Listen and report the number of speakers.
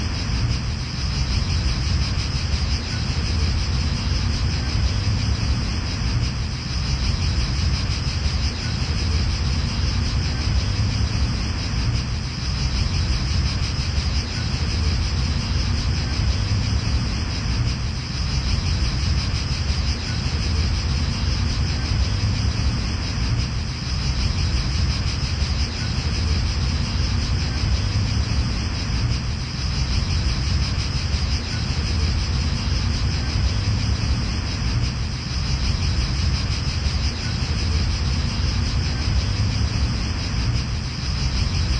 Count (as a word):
zero